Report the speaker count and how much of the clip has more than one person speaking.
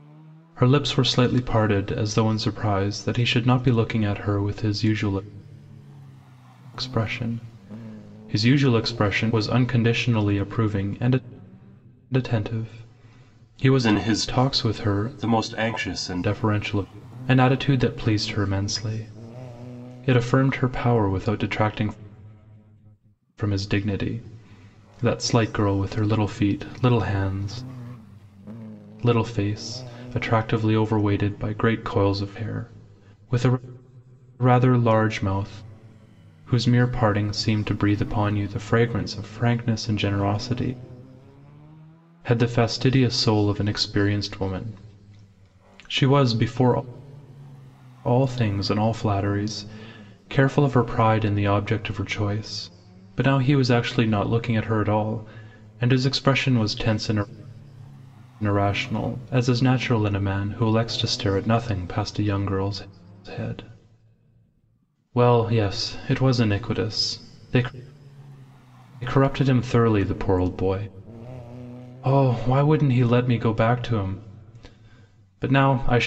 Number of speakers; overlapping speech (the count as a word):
one, no overlap